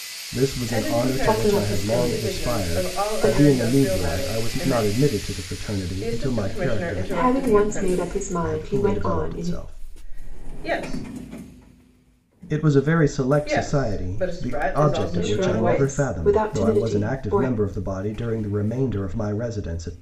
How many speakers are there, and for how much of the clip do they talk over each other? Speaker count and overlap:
3, about 61%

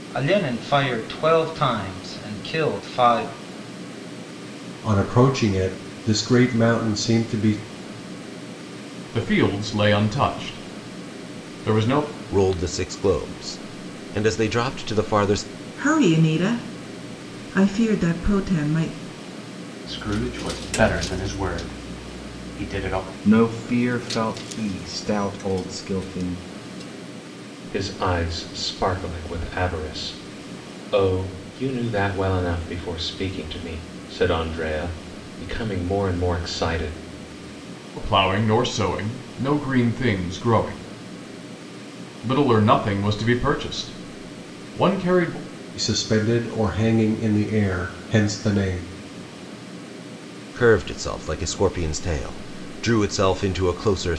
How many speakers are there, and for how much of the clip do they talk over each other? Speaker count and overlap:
8, no overlap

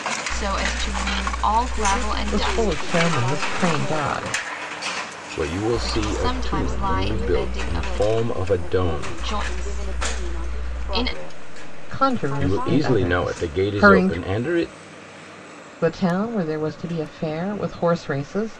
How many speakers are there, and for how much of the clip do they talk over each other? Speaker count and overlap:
4, about 55%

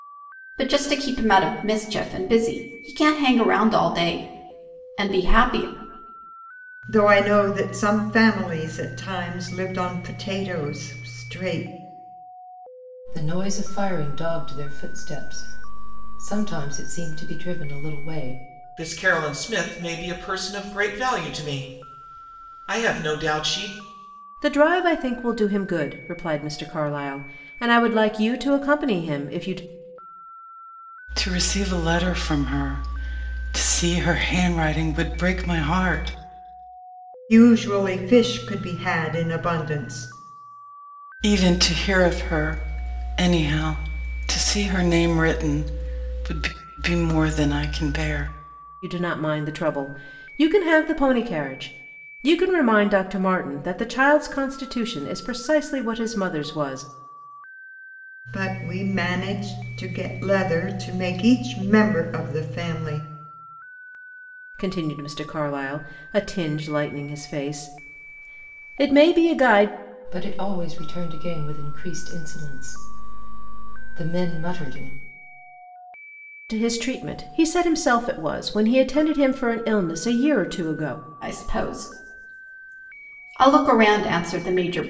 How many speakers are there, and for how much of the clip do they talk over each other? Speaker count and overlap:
6, no overlap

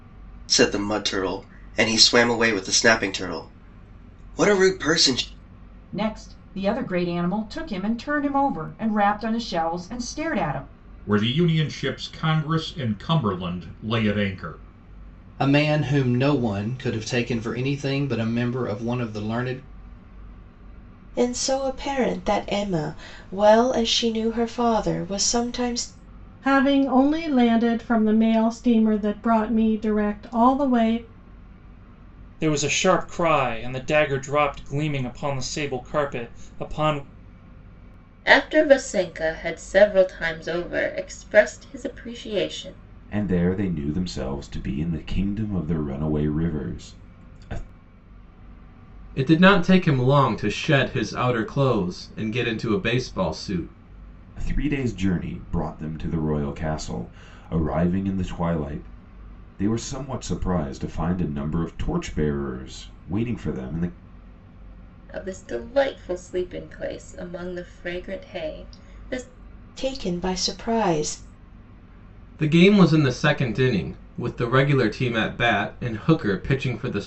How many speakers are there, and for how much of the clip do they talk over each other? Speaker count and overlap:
10, no overlap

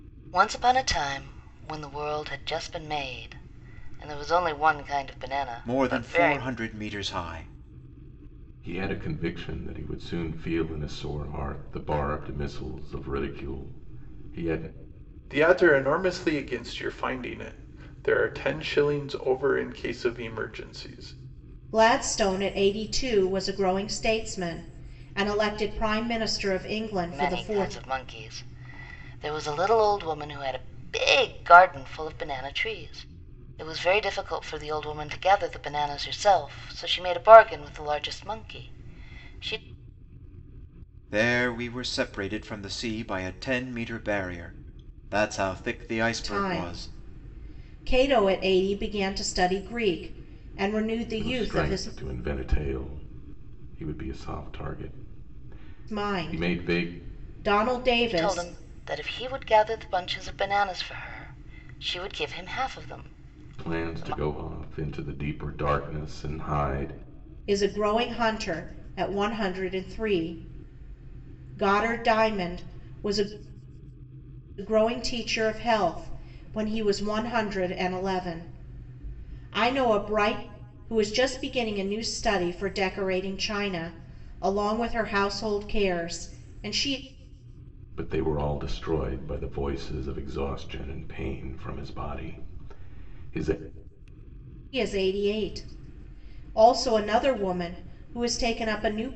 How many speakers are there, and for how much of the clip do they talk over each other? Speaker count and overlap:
5, about 5%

